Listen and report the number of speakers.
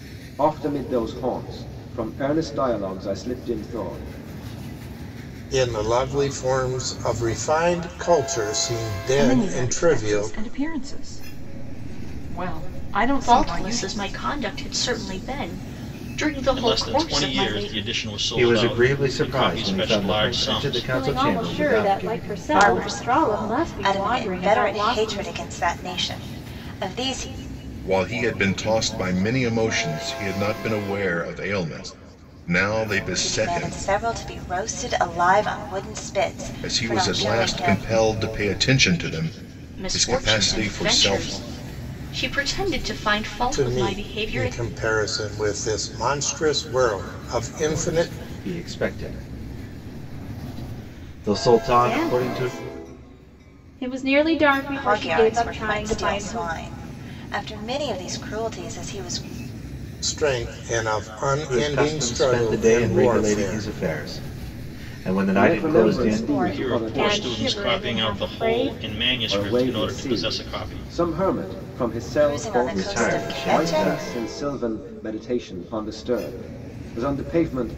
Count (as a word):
nine